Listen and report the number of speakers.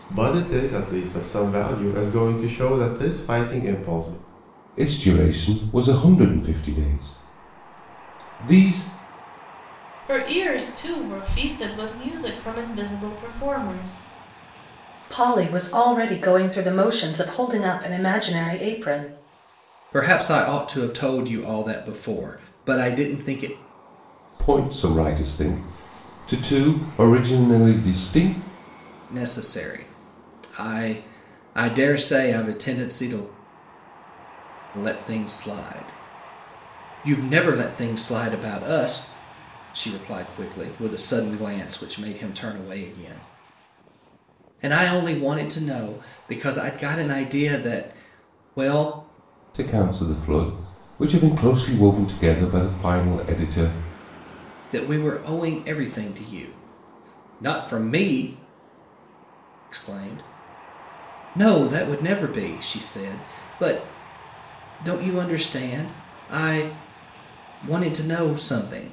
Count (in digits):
5